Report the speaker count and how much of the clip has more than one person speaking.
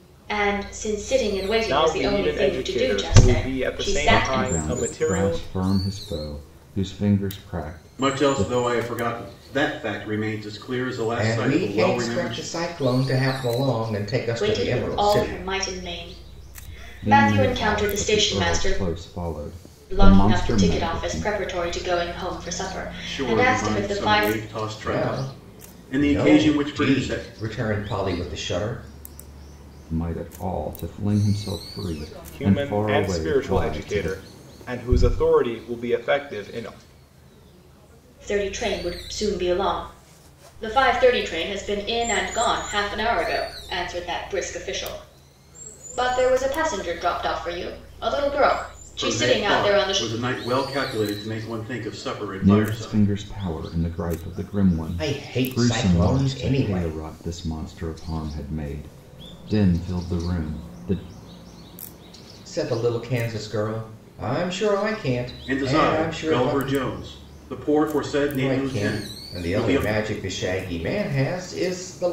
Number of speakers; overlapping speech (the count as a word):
five, about 31%